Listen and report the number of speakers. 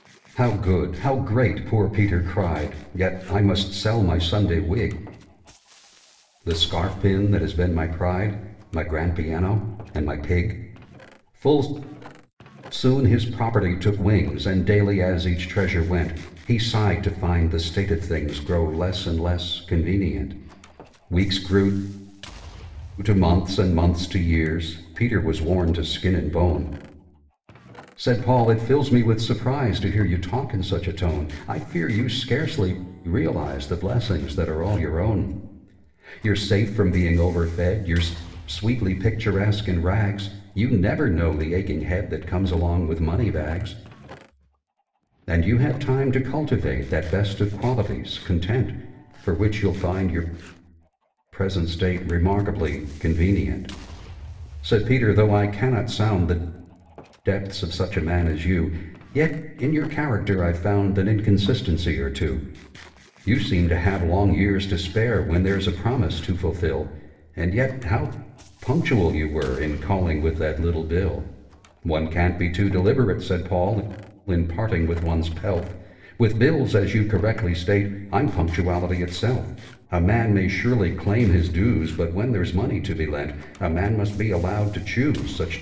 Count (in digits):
1